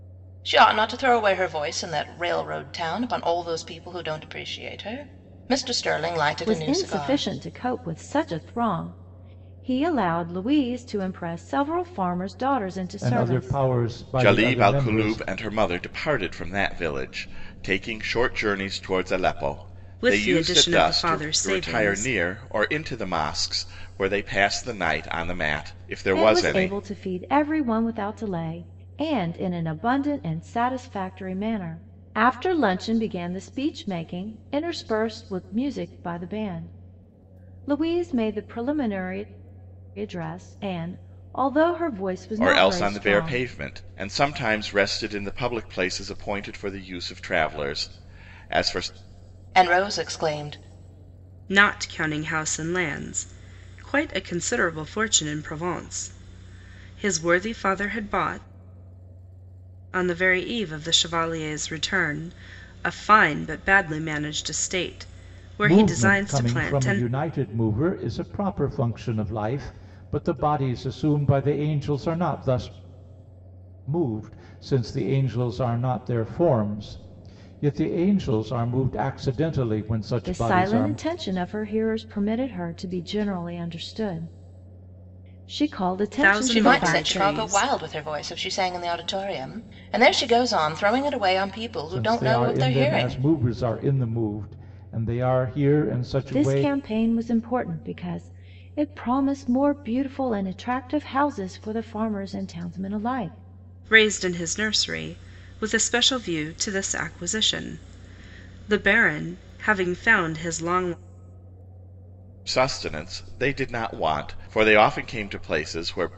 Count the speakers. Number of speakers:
5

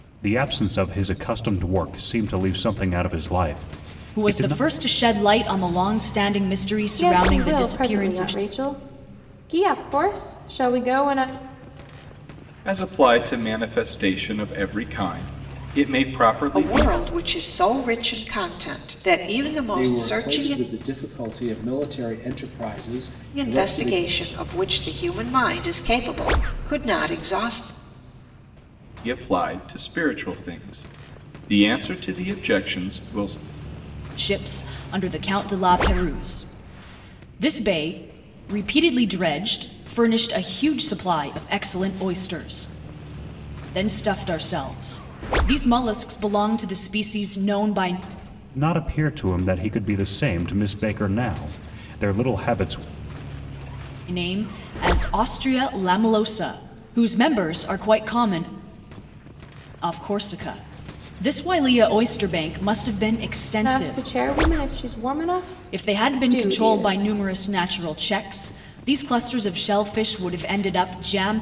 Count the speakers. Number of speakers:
6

